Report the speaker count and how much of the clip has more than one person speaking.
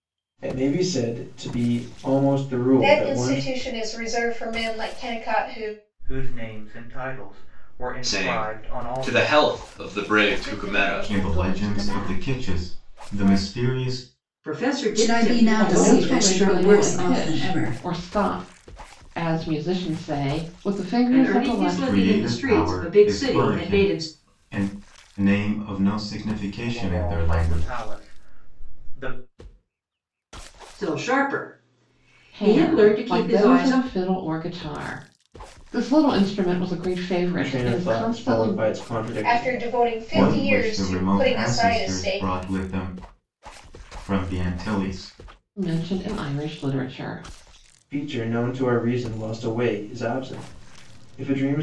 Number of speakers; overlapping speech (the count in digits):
9, about 35%